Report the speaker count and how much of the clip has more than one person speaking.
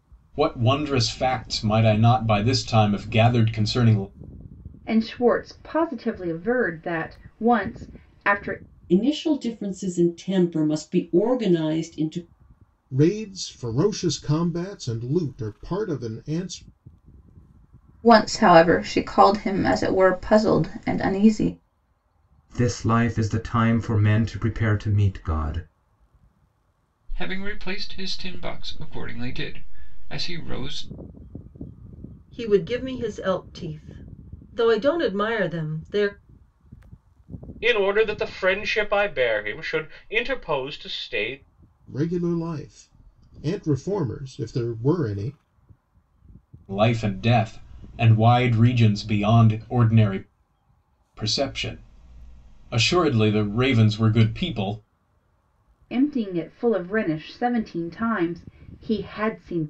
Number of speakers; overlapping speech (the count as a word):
nine, no overlap